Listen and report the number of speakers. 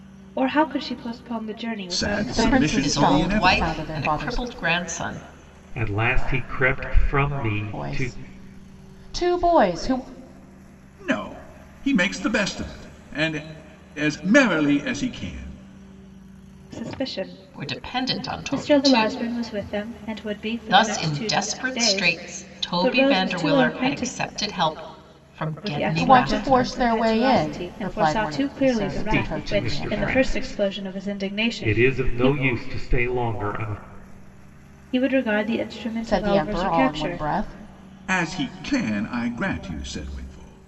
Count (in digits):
5